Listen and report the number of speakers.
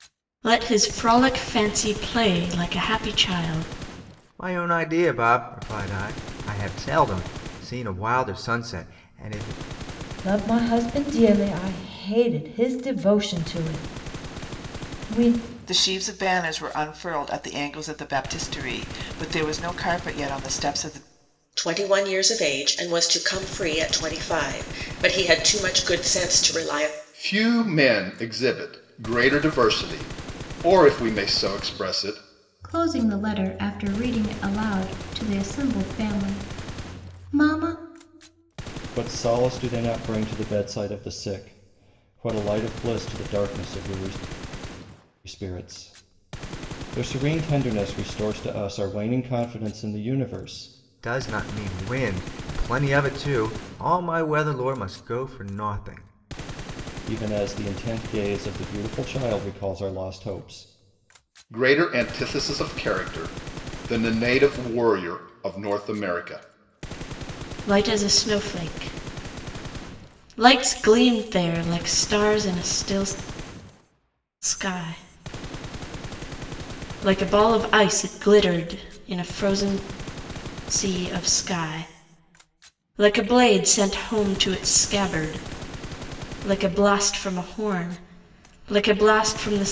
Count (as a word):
eight